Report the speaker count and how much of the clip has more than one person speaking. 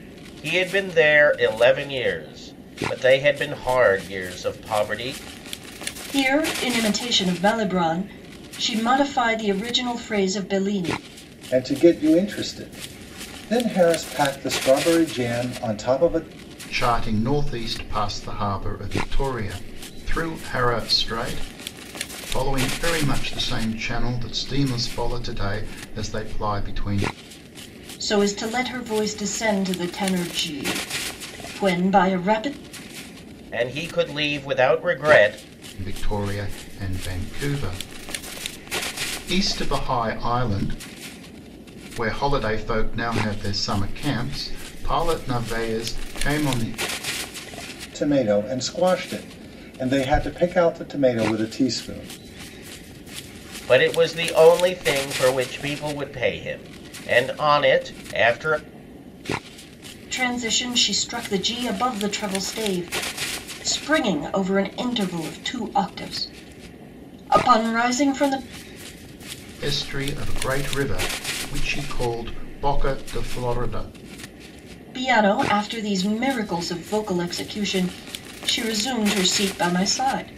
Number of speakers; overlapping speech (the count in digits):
4, no overlap